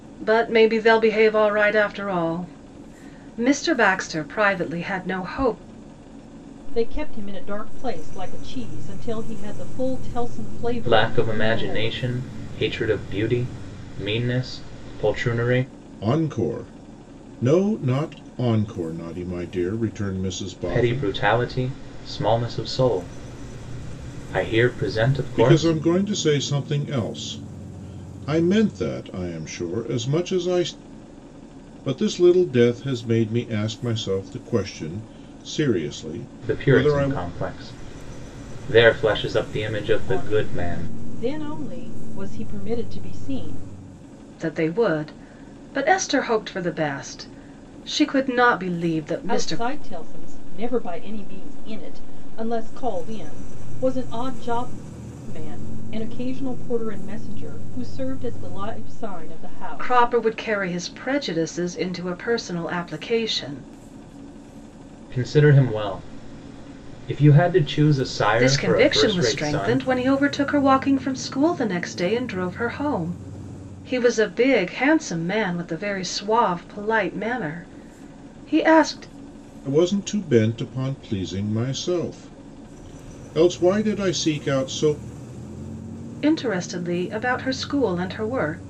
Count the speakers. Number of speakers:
four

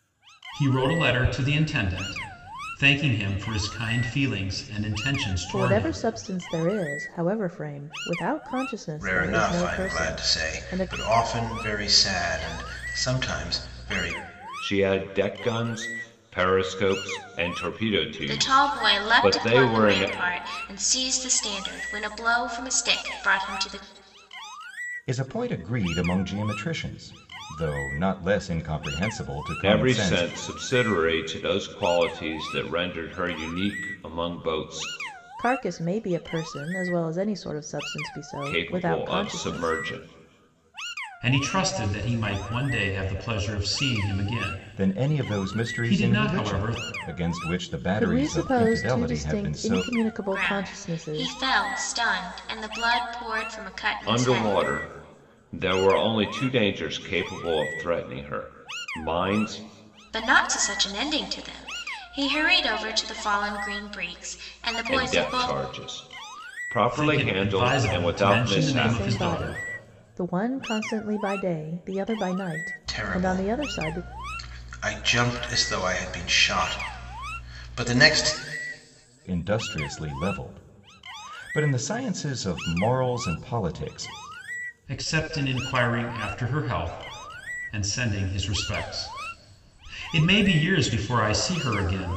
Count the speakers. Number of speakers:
six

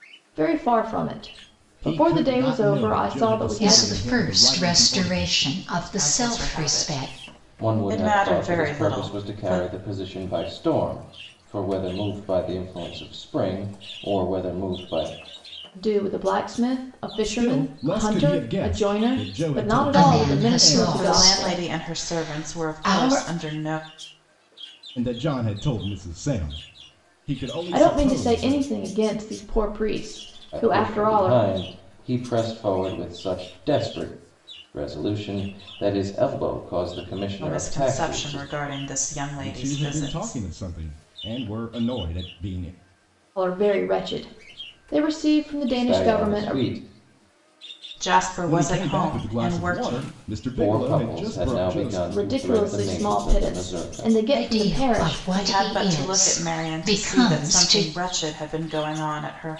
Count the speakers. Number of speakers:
five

